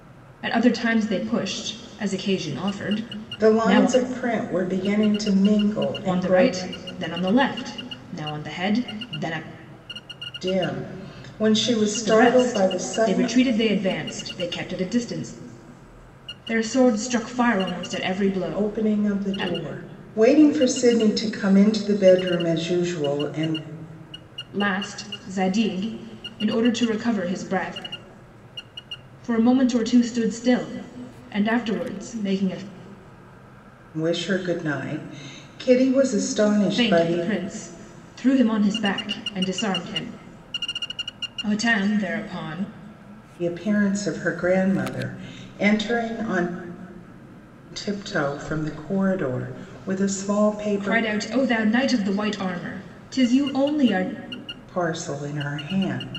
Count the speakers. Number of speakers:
2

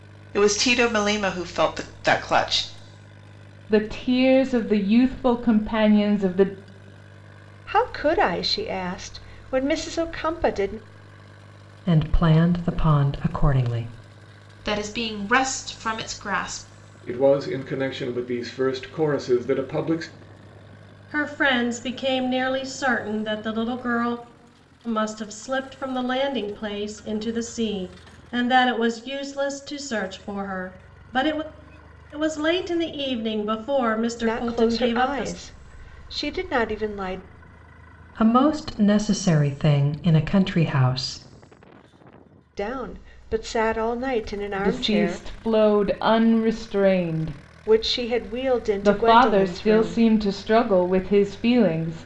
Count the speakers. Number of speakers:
7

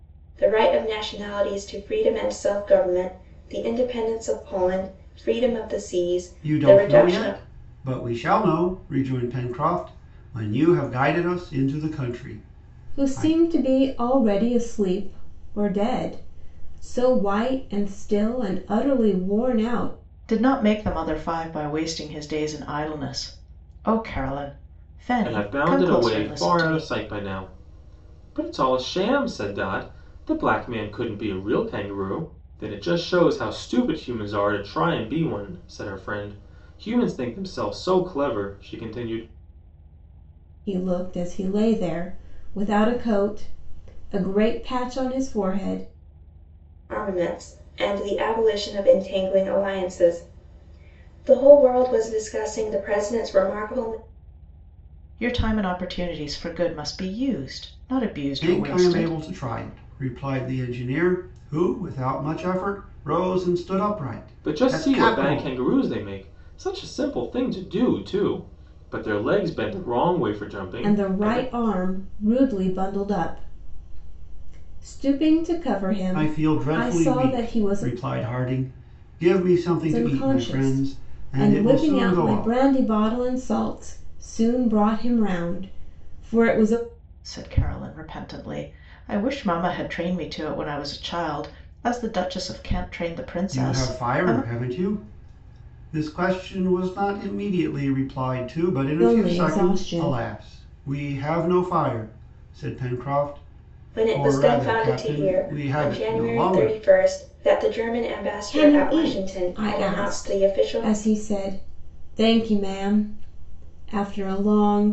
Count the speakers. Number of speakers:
5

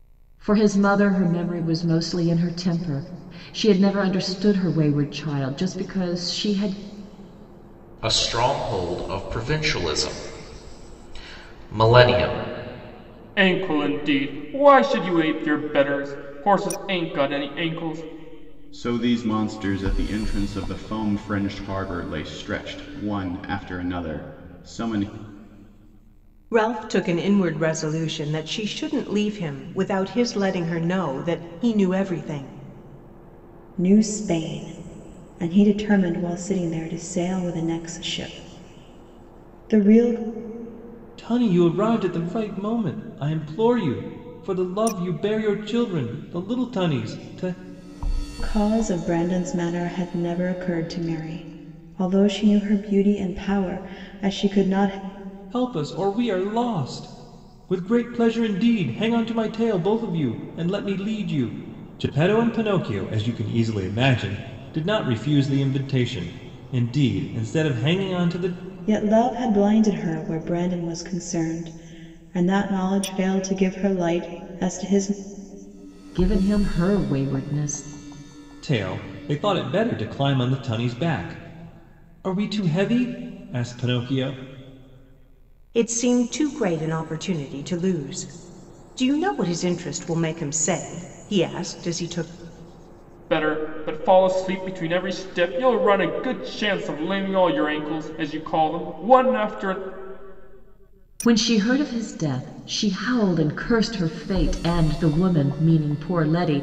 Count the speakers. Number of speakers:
7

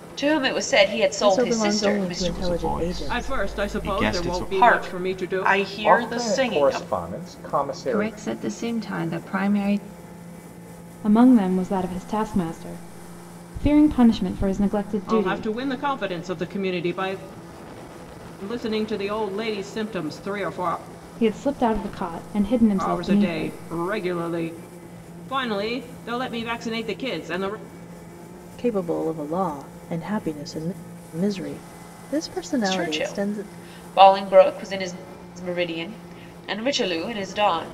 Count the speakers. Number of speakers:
8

